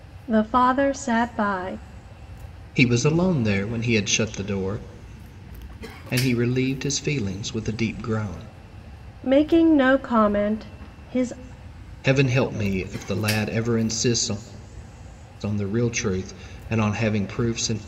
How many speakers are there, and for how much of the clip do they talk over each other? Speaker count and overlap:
two, no overlap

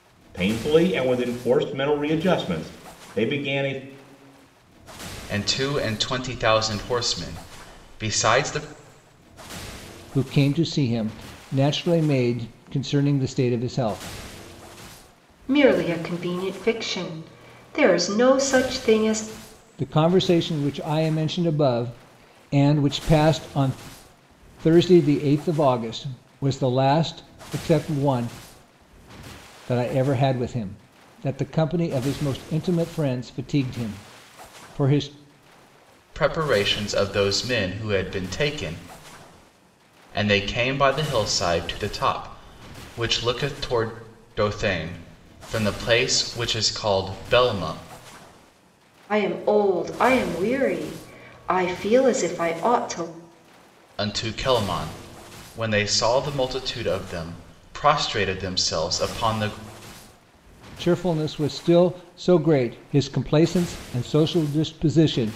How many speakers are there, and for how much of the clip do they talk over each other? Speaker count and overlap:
four, no overlap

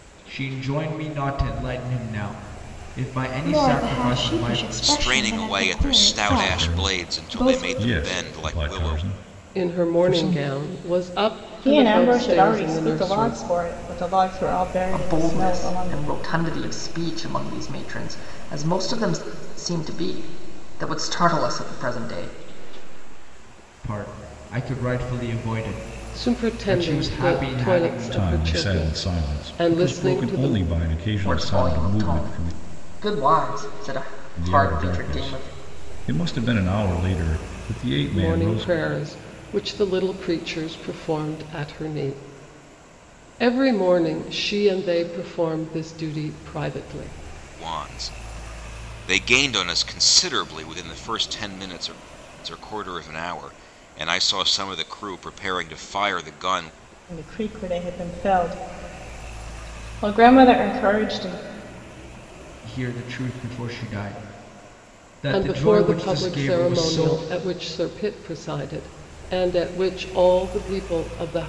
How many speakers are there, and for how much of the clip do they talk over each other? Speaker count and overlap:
seven, about 26%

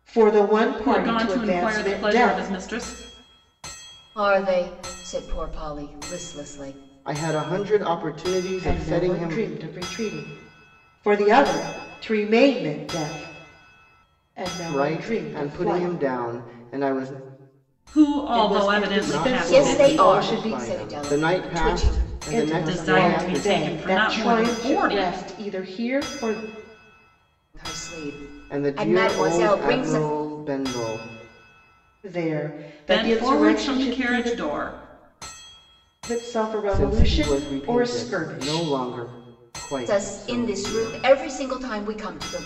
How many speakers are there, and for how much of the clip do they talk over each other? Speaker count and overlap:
four, about 39%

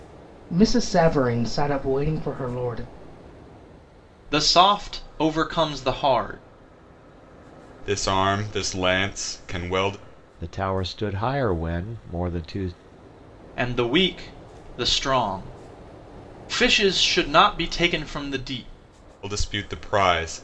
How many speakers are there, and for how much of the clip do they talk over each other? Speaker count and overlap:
four, no overlap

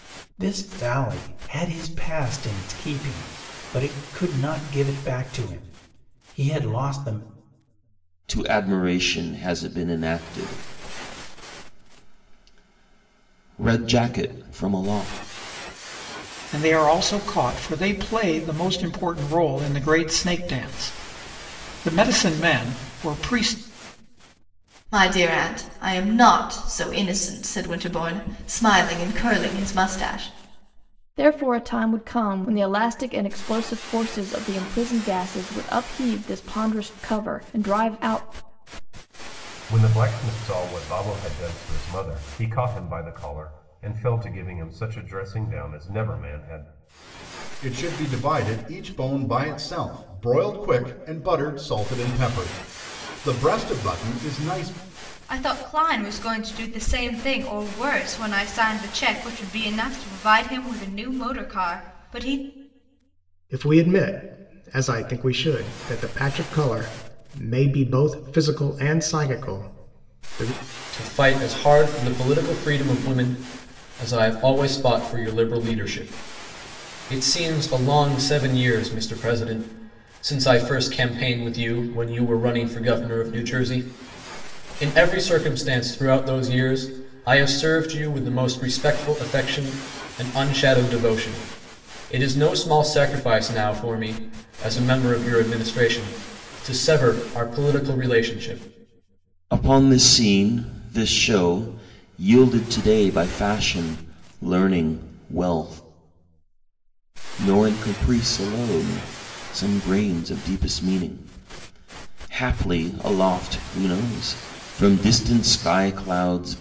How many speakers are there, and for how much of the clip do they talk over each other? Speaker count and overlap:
ten, no overlap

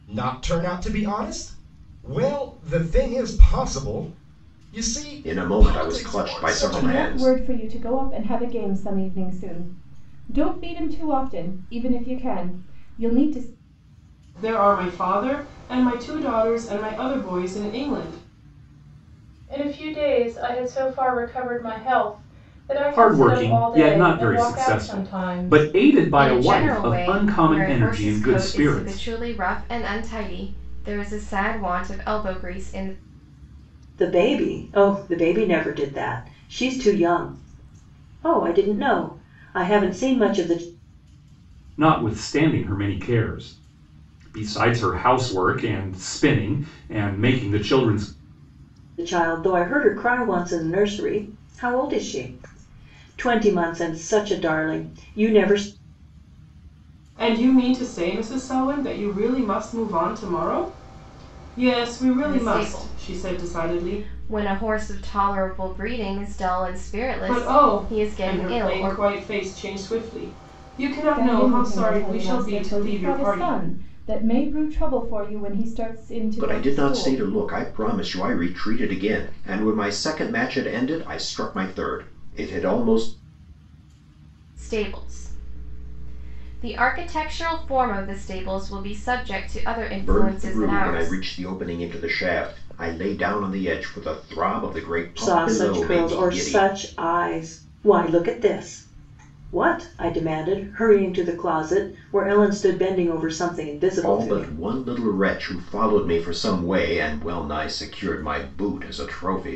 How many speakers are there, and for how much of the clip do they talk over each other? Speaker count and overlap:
eight, about 16%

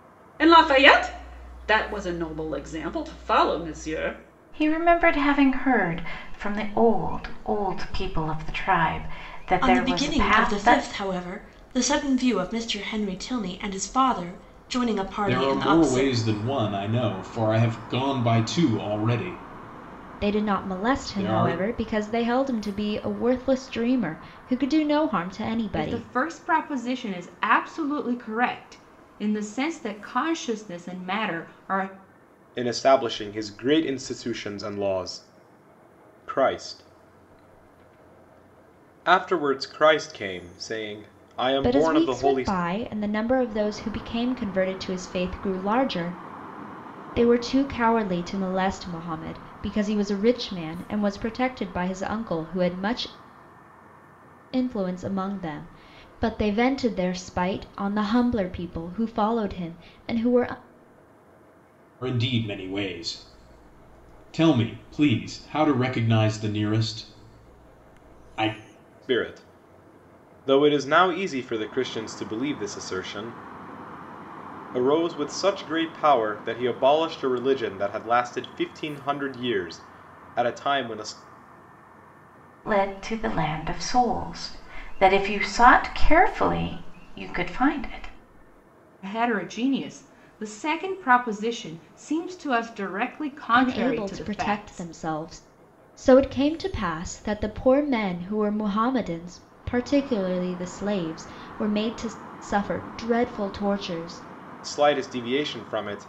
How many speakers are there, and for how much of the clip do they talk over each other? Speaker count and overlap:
seven, about 6%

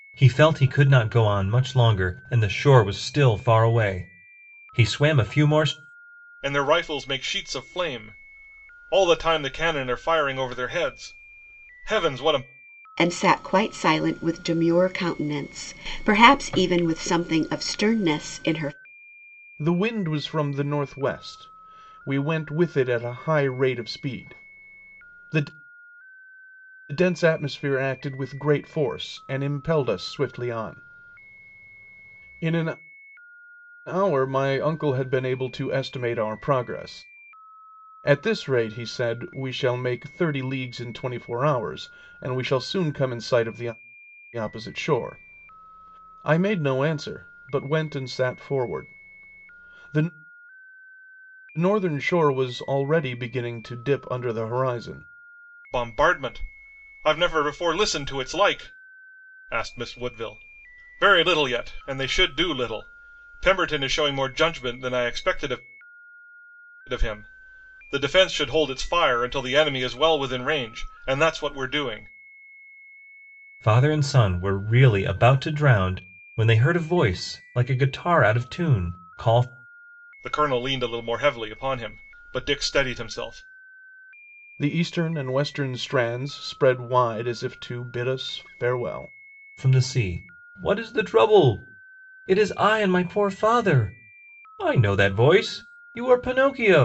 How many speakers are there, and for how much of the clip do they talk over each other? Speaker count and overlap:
four, no overlap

